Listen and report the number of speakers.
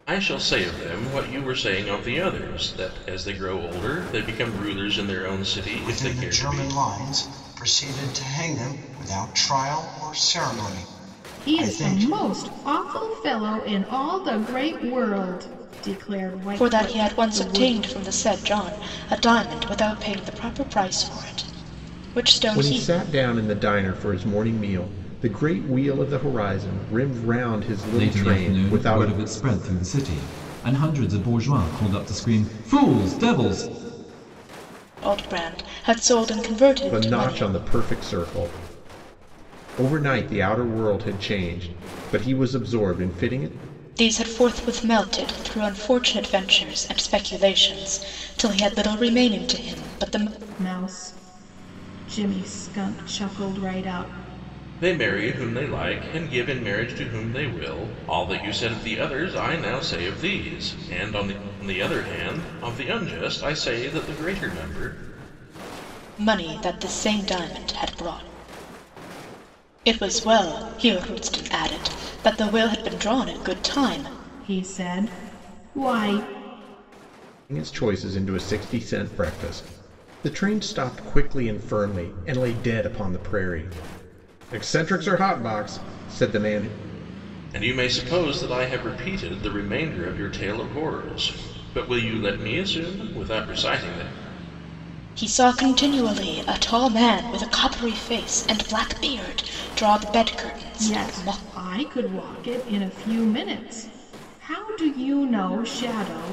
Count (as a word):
six